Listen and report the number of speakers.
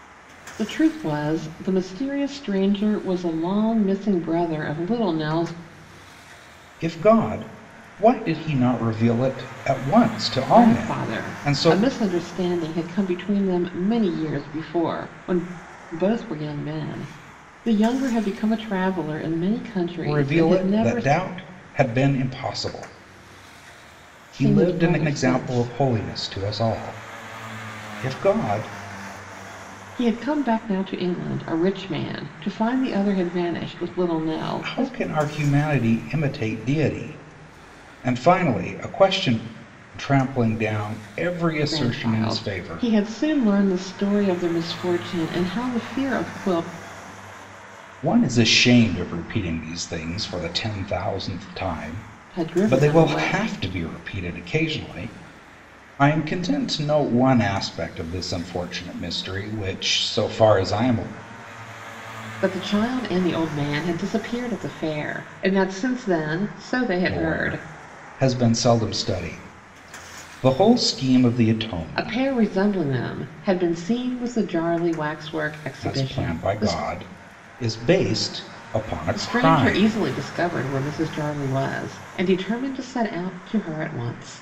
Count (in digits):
2